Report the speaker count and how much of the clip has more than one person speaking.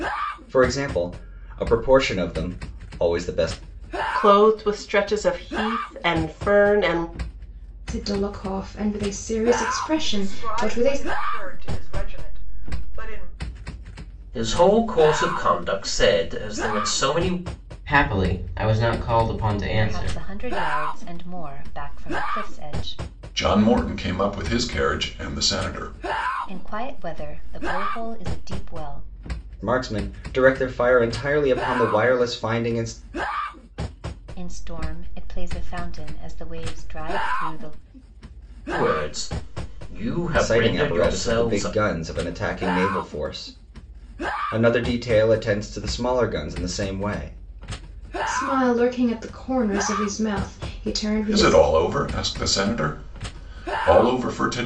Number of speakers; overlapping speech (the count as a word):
eight, about 6%